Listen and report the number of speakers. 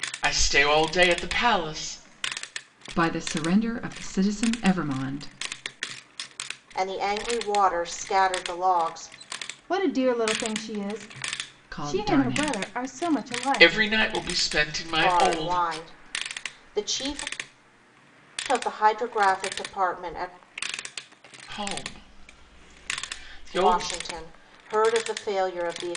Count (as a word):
four